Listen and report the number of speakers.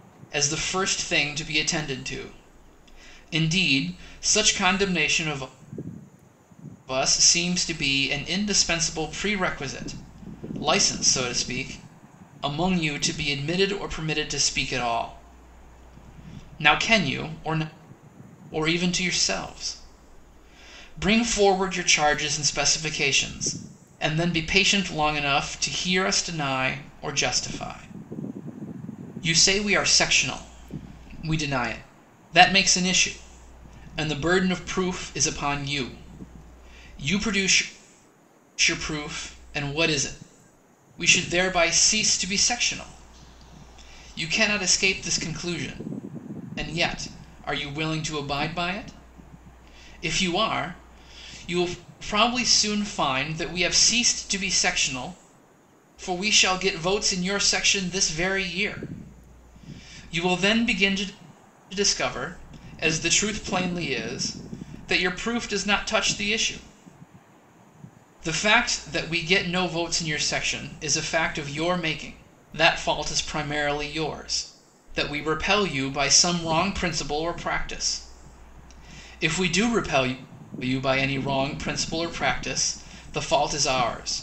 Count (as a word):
one